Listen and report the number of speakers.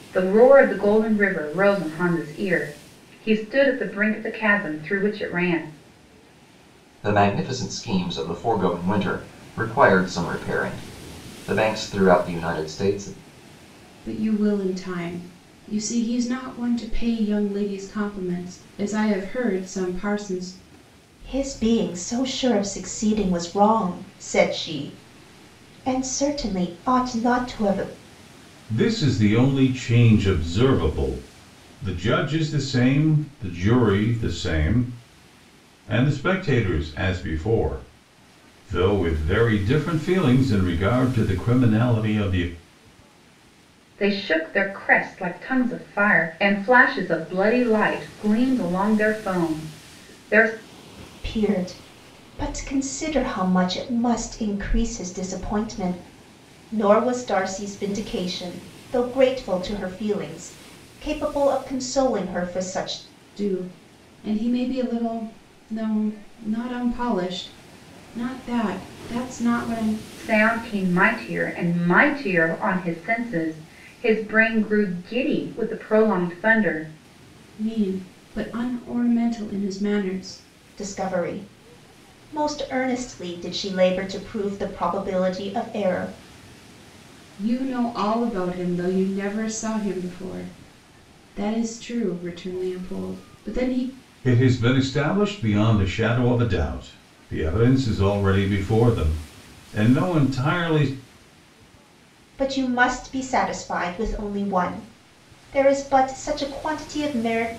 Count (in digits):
5